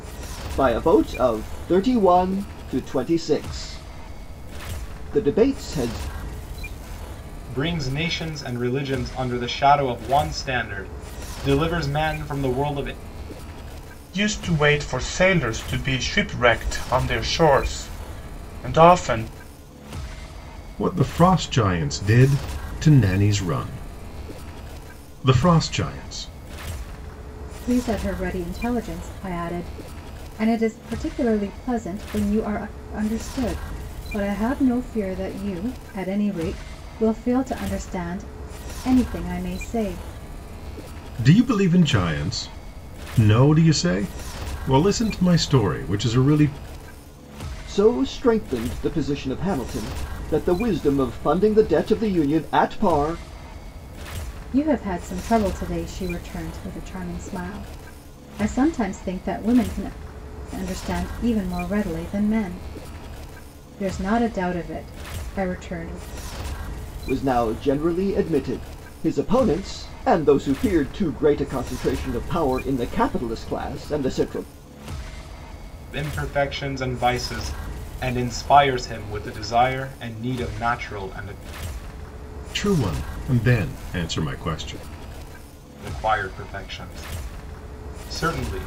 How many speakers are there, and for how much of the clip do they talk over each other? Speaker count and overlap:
5, no overlap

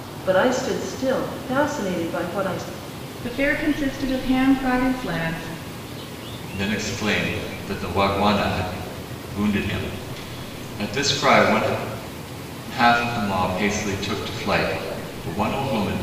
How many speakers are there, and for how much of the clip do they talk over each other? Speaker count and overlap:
3, no overlap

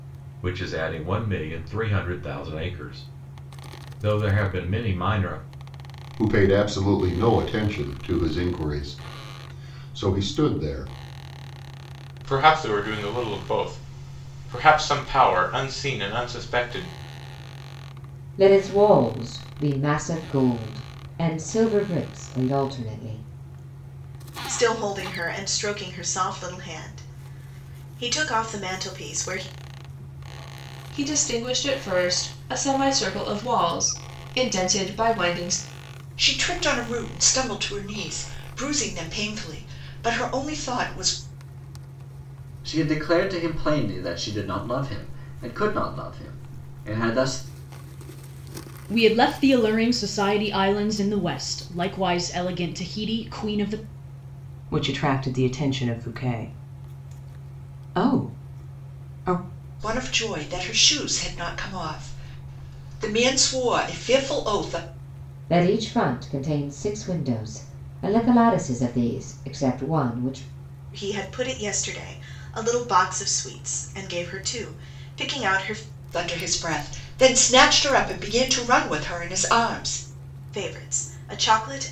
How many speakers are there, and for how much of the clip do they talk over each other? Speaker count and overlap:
10, no overlap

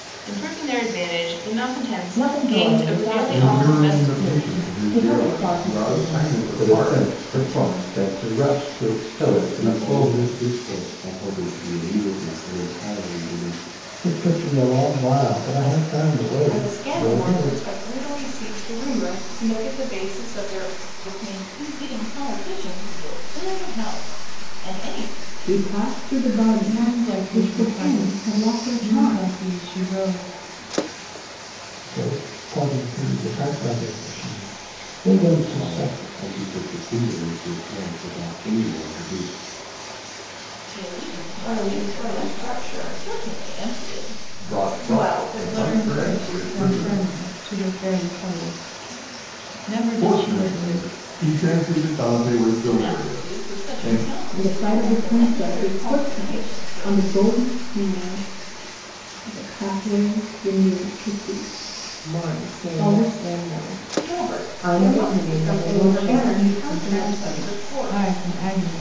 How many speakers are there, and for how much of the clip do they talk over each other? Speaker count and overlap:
10, about 40%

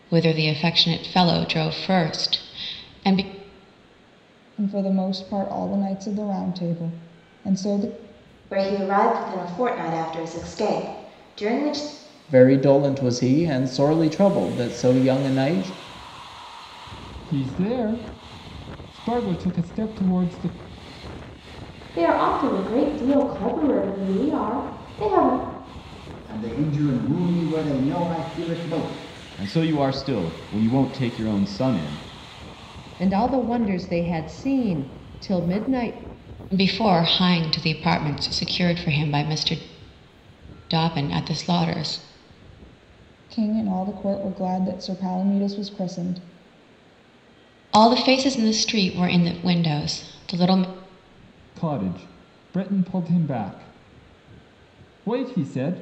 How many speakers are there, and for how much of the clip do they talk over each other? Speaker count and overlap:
9, no overlap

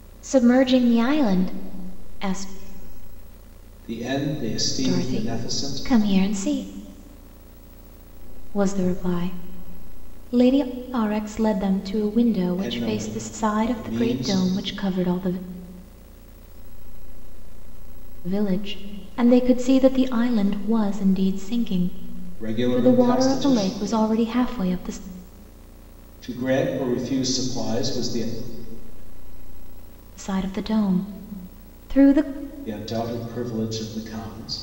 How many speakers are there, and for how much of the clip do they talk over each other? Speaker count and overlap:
3, about 39%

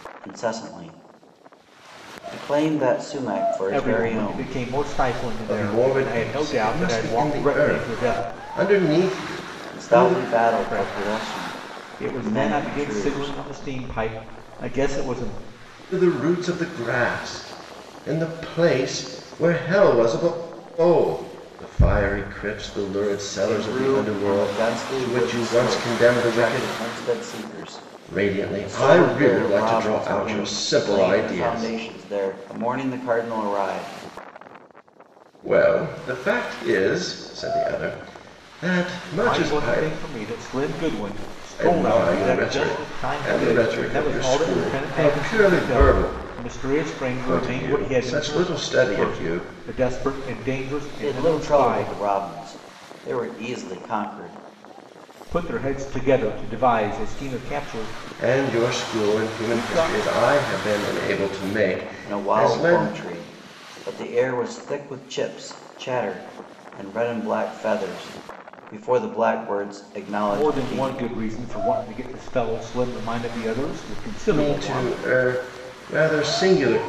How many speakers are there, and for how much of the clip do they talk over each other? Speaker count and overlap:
3, about 34%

